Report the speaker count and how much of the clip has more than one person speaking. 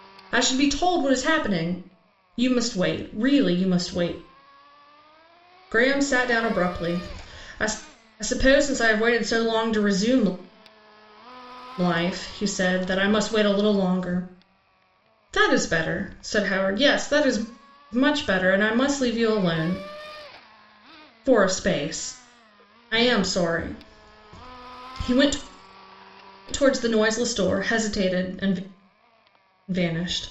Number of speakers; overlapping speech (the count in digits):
1, no overlap